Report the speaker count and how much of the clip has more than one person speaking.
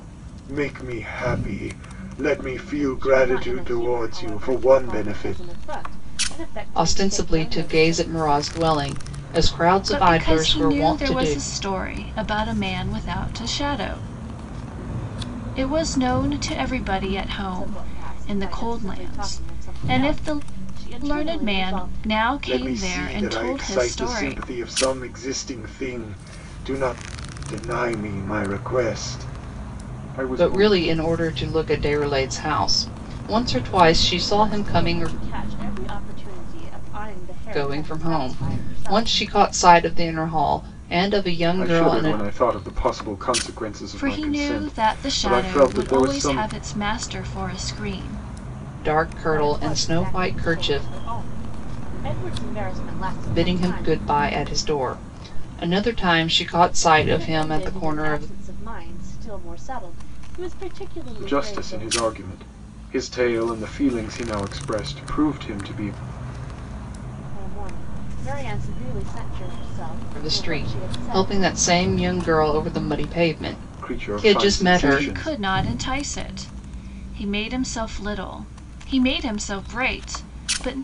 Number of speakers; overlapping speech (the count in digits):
4, about 32%